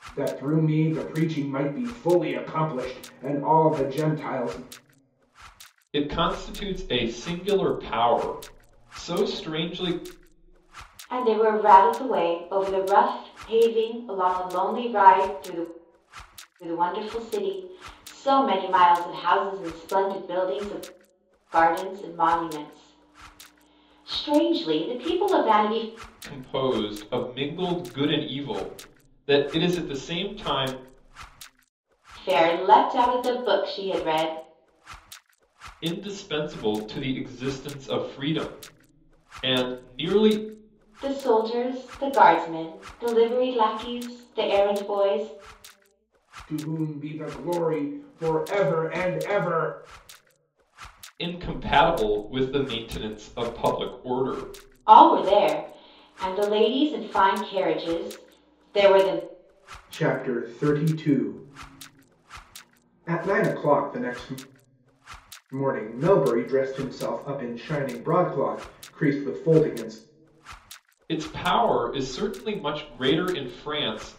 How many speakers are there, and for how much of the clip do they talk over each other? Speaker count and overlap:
three, no overlap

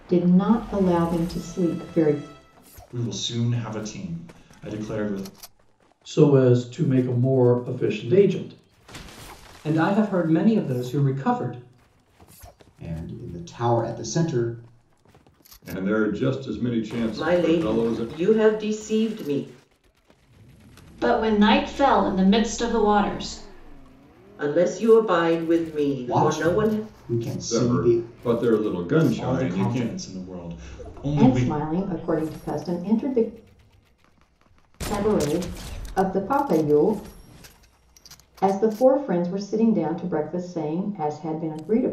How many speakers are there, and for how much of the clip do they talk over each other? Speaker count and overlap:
eight, about 8%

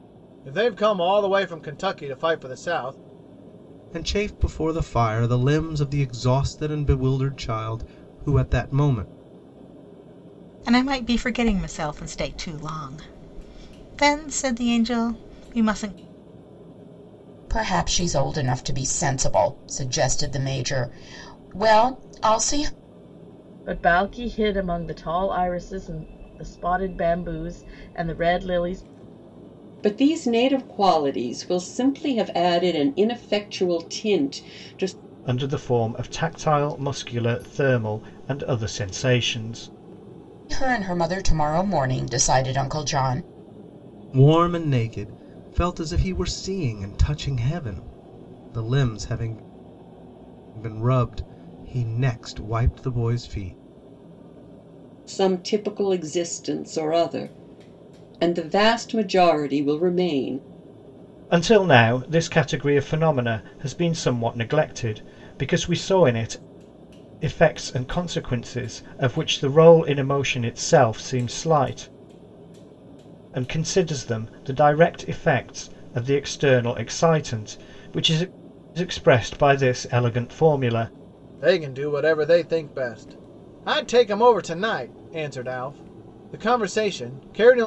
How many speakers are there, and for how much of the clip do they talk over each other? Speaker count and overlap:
seven, no overlap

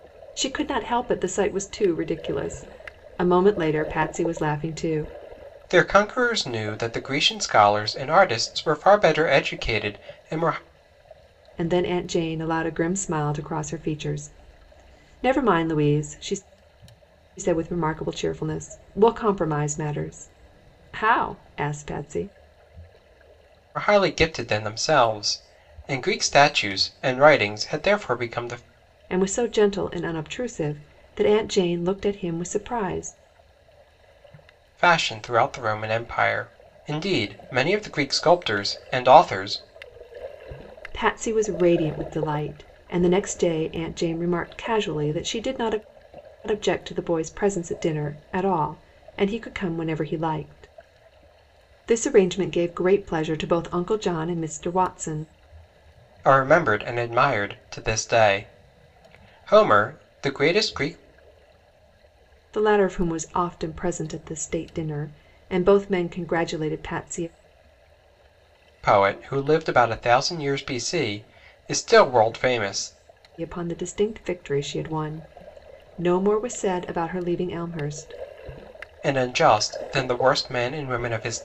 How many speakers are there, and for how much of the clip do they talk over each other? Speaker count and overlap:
two, no overlap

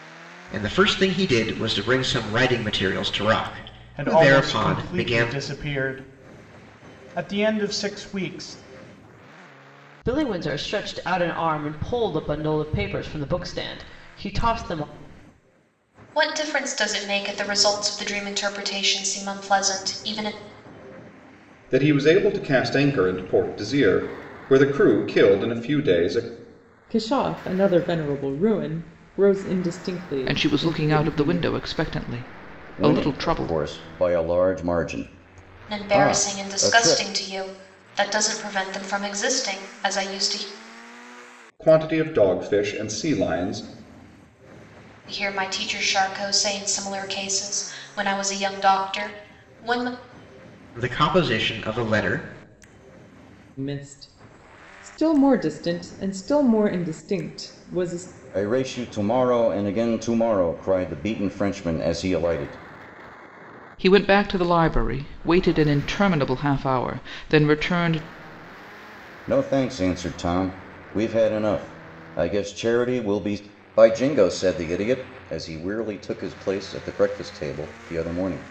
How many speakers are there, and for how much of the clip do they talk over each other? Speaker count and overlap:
eight, about 6%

